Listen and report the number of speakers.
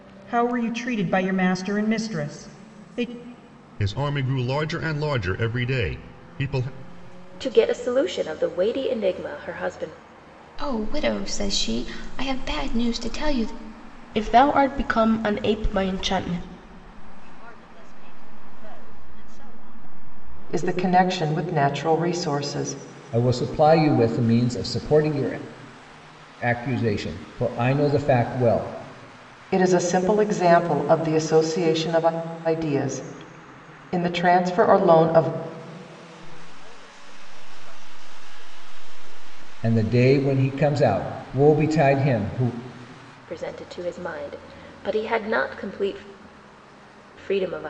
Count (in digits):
8